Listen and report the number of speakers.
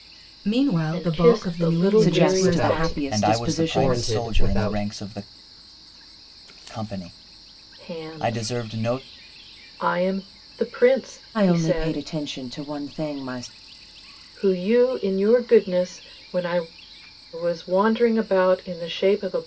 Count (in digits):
5